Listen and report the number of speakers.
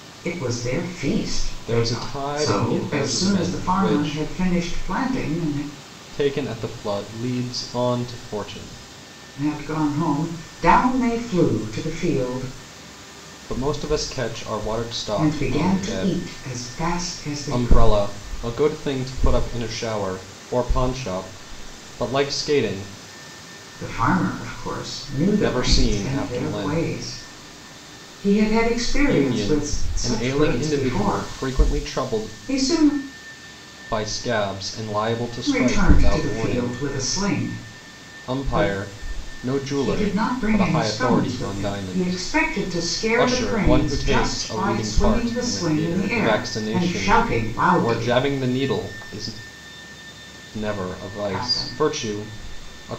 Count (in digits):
2